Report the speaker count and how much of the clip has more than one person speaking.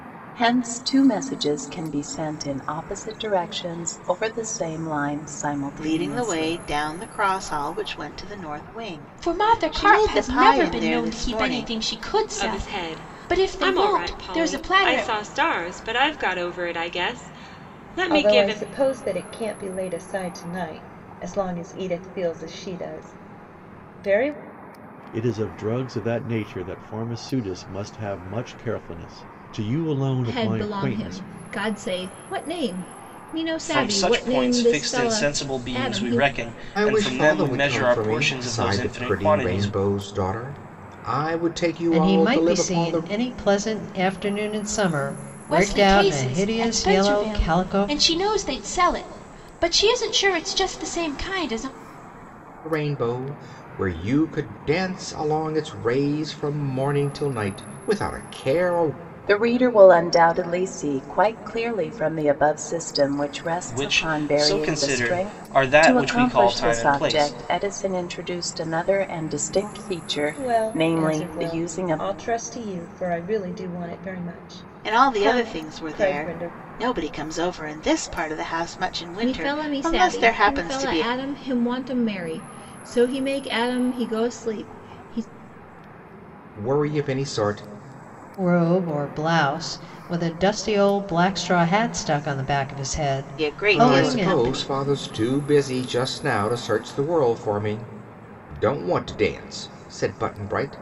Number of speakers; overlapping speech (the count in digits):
10, about 27%